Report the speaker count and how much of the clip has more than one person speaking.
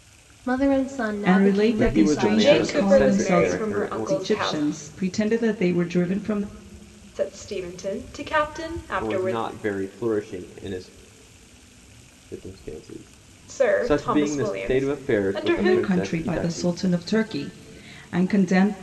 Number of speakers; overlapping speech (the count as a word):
four, about 39%